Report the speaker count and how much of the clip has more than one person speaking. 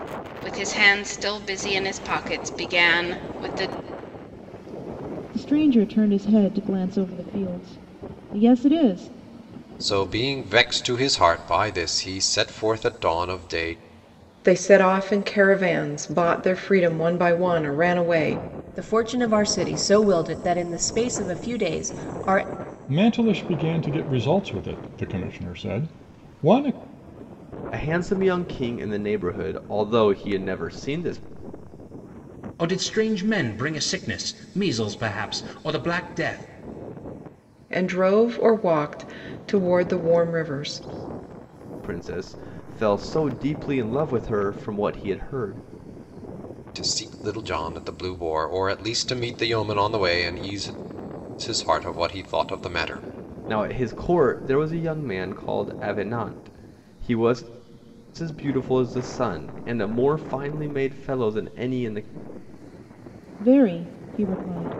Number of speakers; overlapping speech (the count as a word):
eight, no overlap